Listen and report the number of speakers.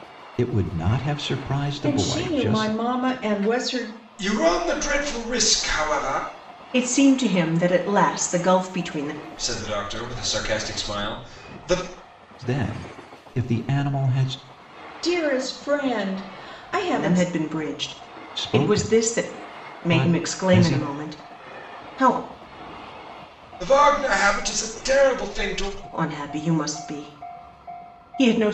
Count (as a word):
four